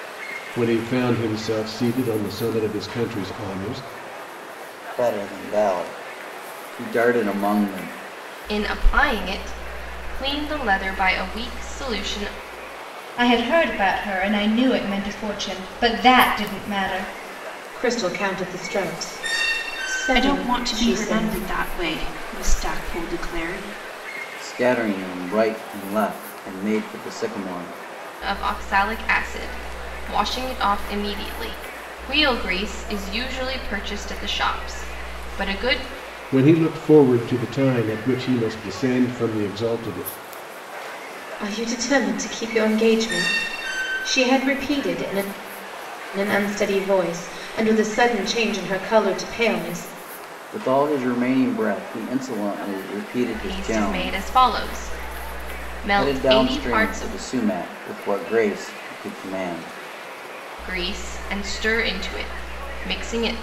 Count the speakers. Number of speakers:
6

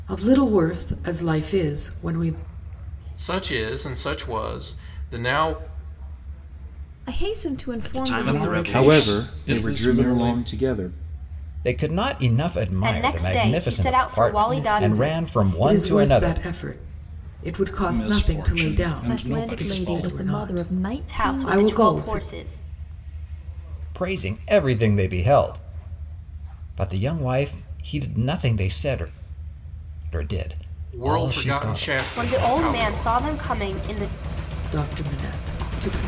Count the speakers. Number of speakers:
8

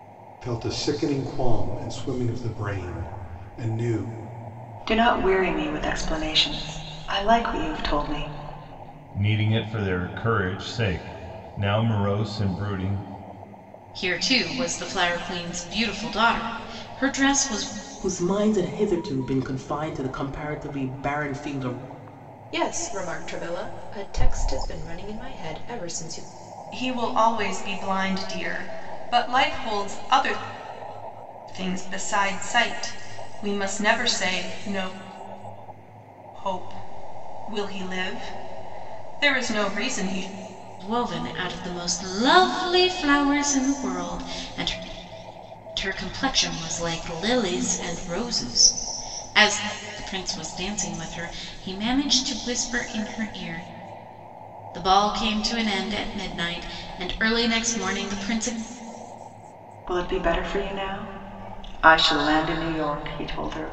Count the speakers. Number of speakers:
7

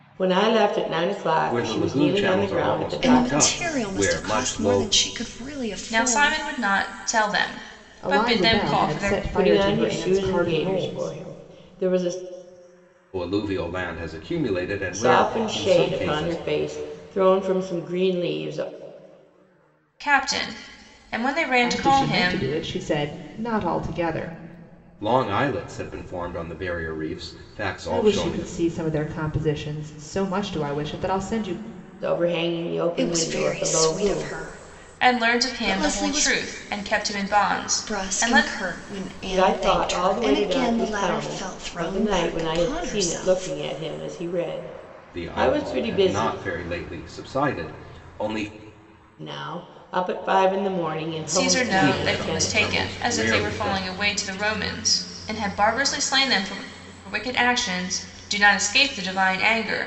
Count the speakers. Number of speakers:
5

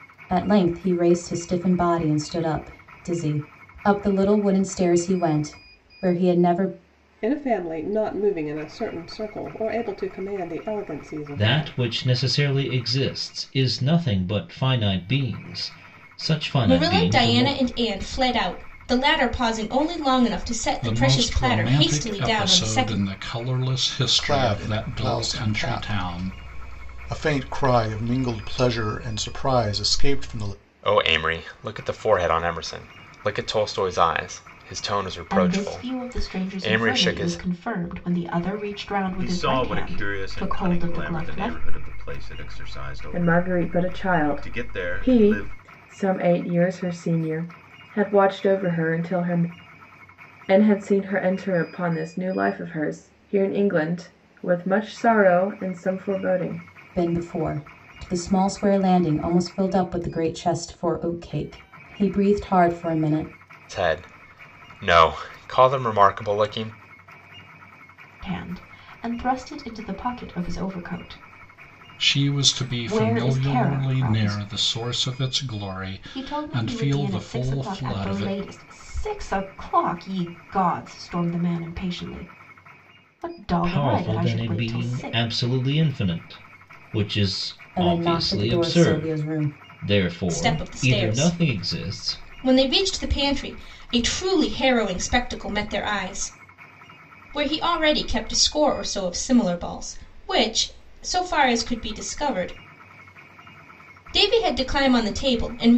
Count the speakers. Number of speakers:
10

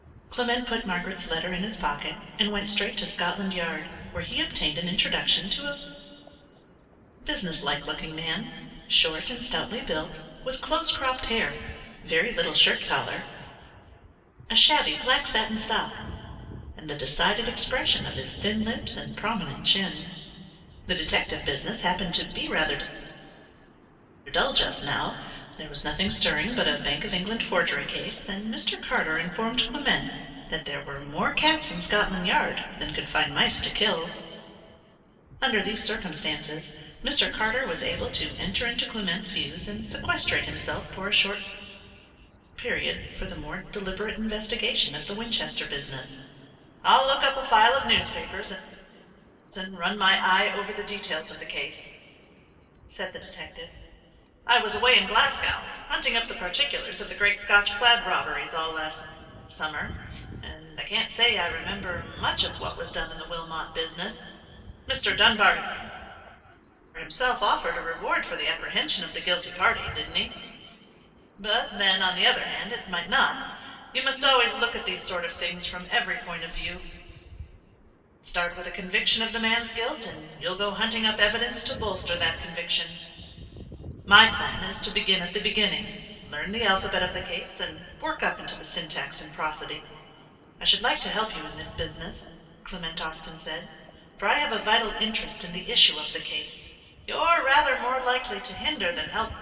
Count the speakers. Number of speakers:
1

